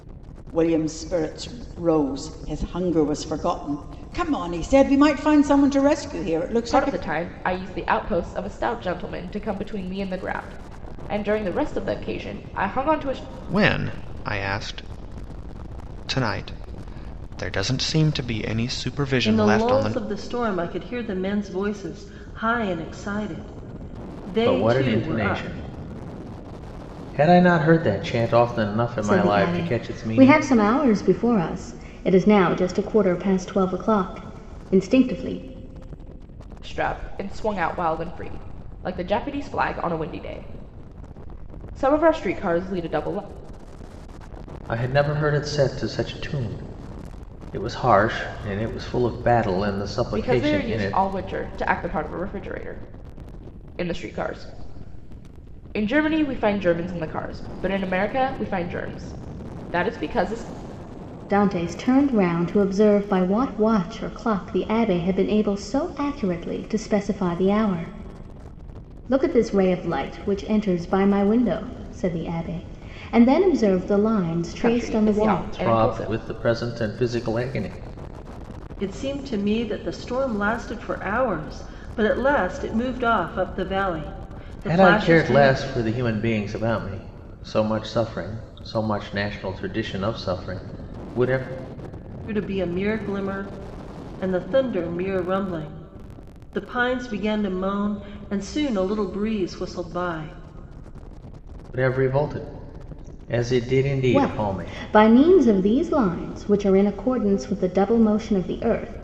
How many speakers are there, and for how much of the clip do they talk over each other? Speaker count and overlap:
6, about 7%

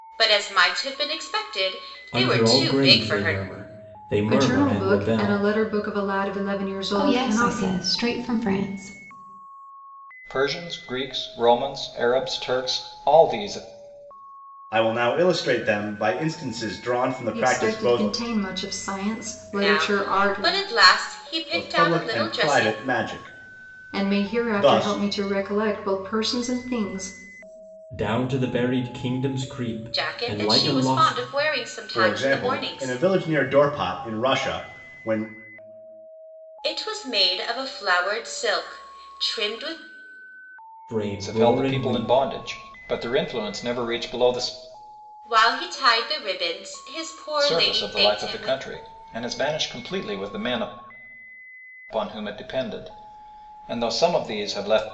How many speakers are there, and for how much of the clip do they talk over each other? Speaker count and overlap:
6, about 22%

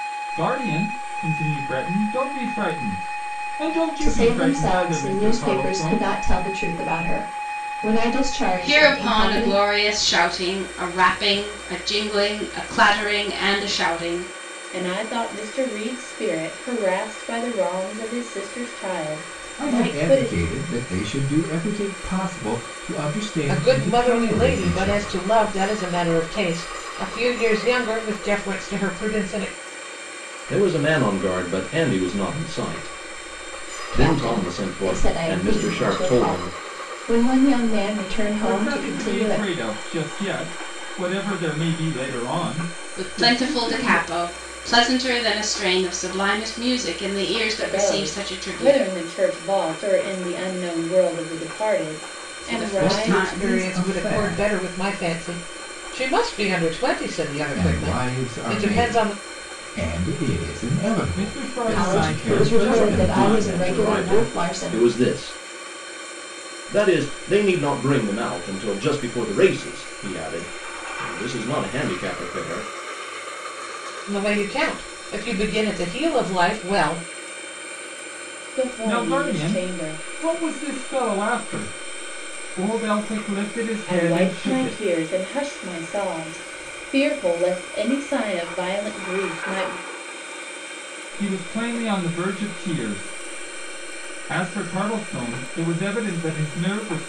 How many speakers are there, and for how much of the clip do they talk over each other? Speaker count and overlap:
7, about 23%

